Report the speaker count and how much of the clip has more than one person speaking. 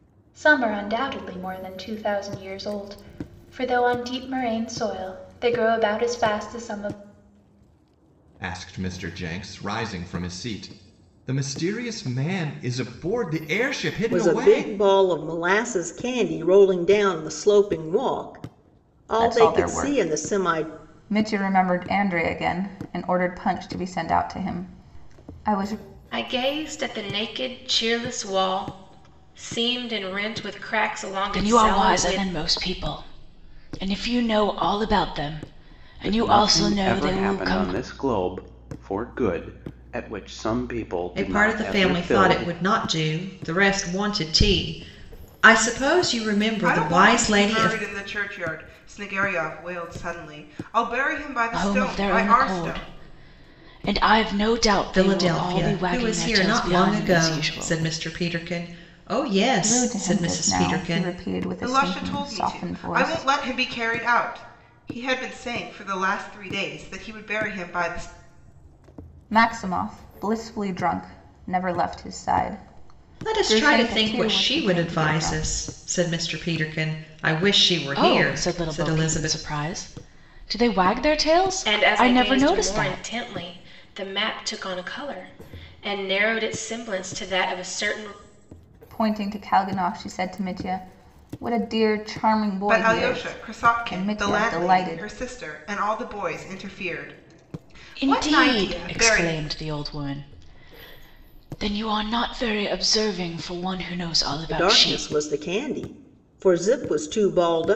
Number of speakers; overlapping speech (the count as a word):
nine, about 23%